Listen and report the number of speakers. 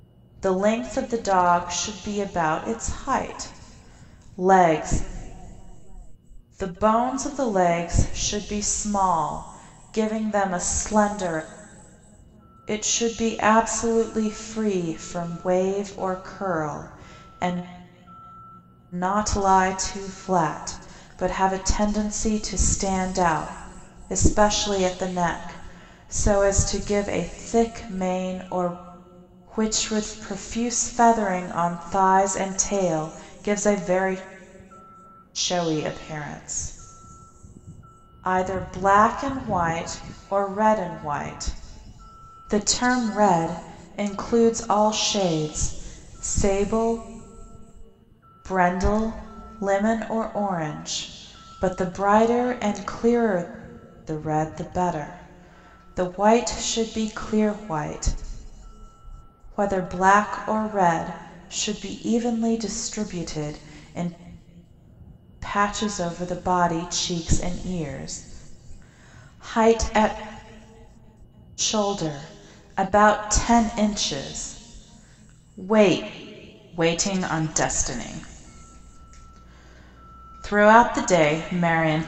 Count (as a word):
one